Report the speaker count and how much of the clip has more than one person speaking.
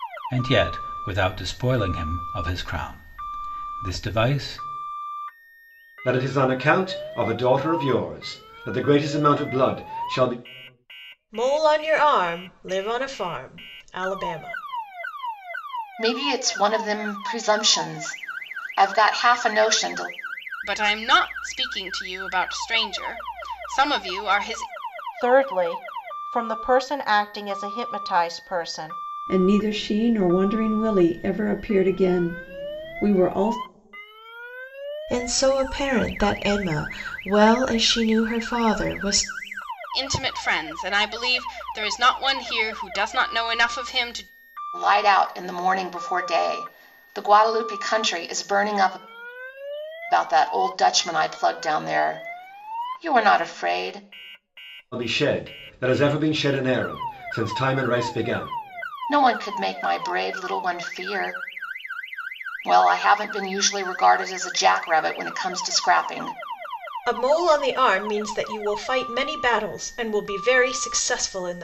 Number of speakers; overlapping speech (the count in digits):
8, no overlap